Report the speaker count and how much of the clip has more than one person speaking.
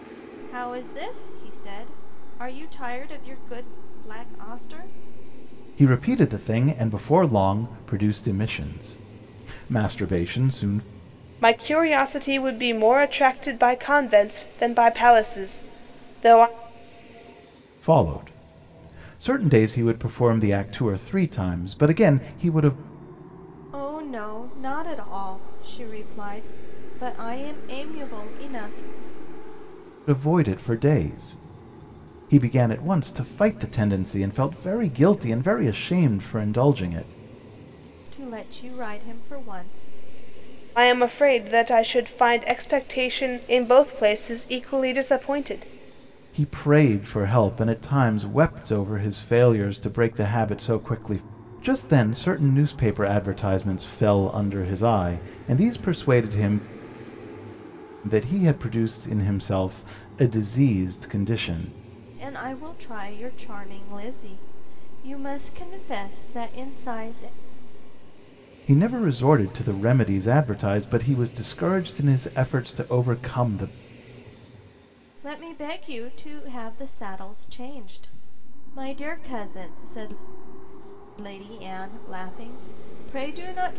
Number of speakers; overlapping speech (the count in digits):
3, no overlap